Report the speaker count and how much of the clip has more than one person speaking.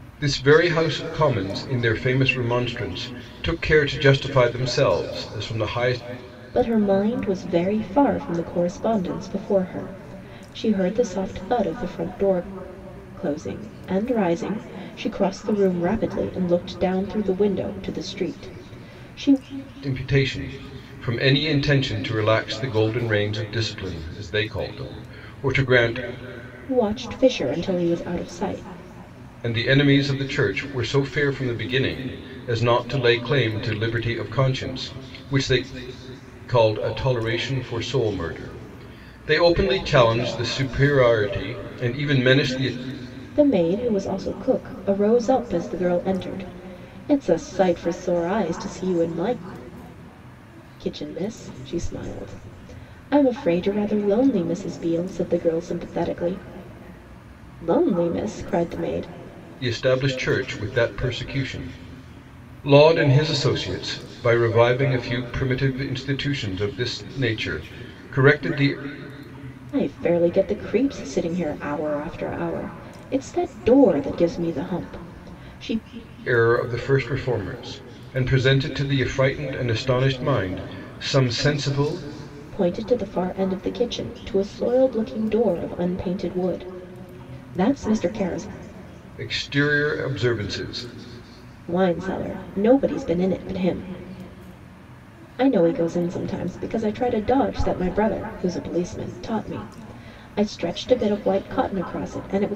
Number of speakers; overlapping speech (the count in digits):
2, no overlap